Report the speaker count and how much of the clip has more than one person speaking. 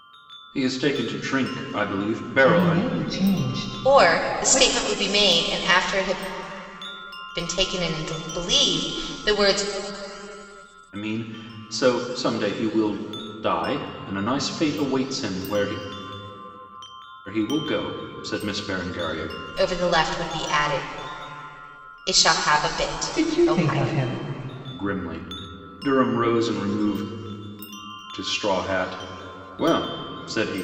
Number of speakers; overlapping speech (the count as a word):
three, about 7%